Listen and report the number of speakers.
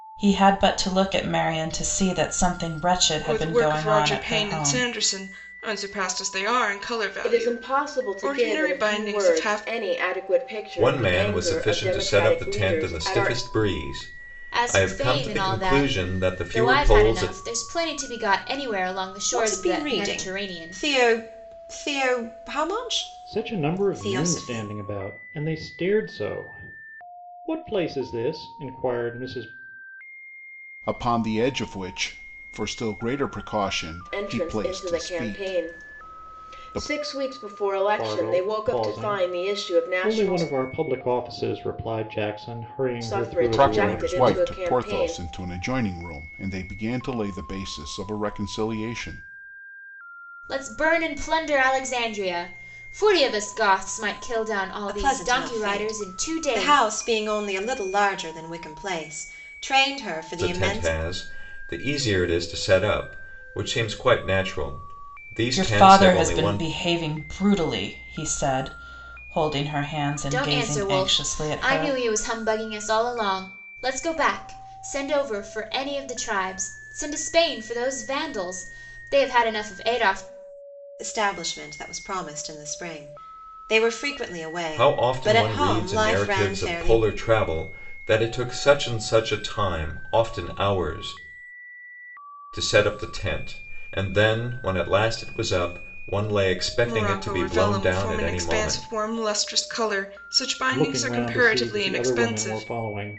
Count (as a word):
eight